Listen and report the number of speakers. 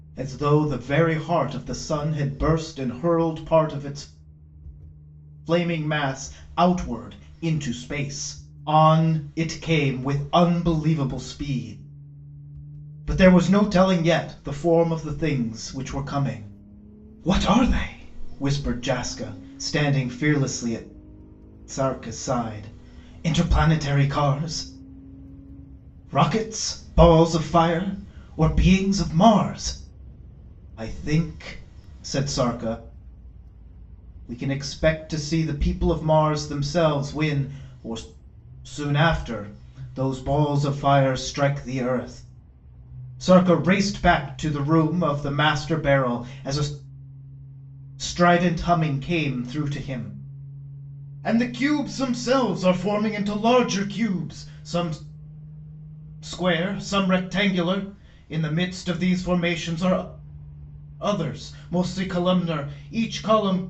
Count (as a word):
one